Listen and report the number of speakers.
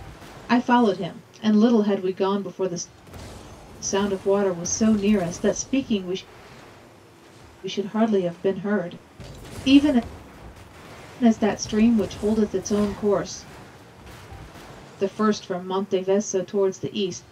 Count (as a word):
one